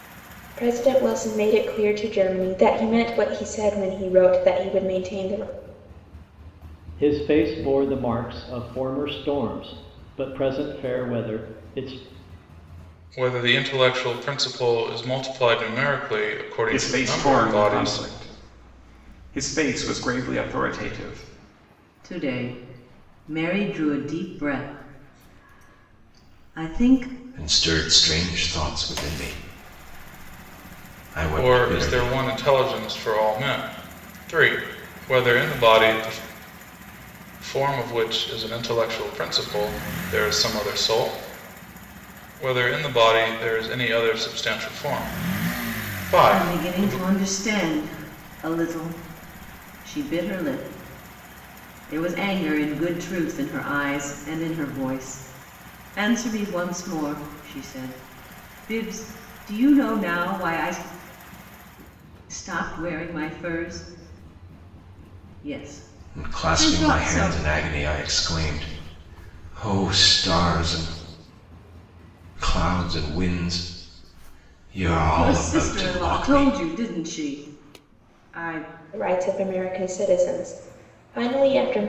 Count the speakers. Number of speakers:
6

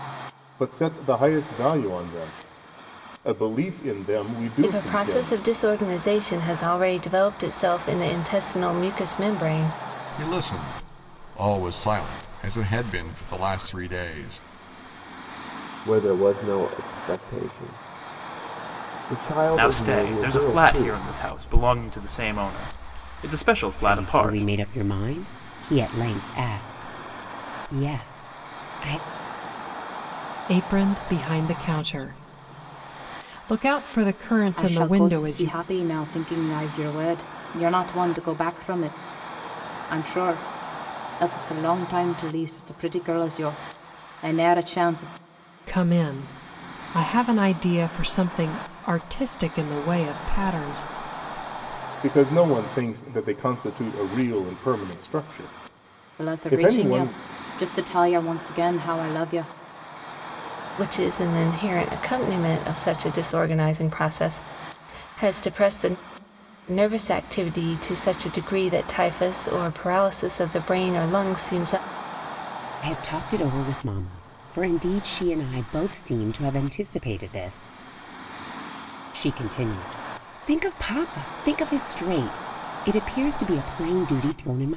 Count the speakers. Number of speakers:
8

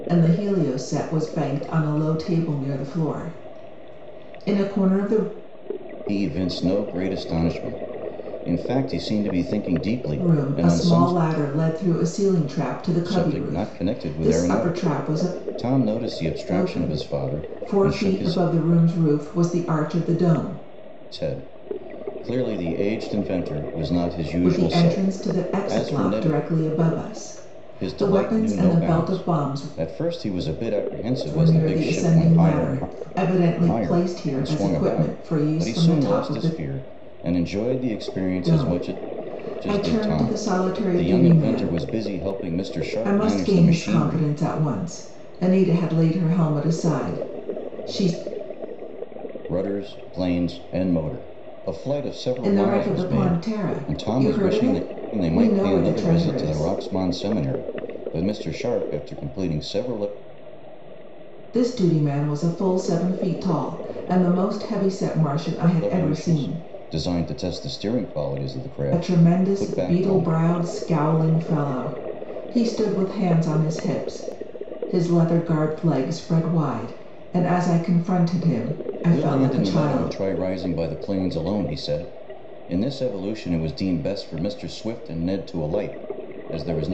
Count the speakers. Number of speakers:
2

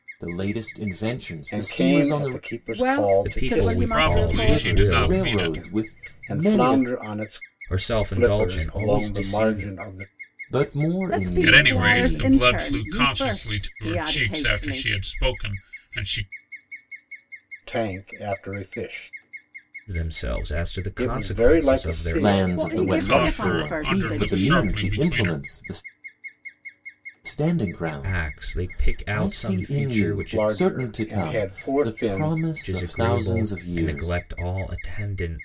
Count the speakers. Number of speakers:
5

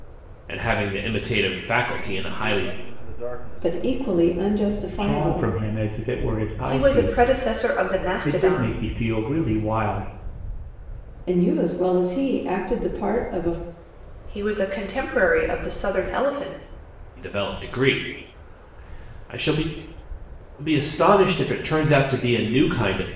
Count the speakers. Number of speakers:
5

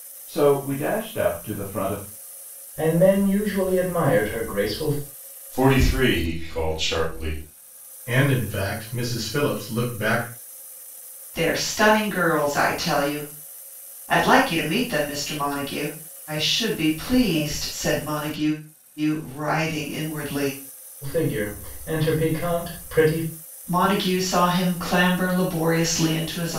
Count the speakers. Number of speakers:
5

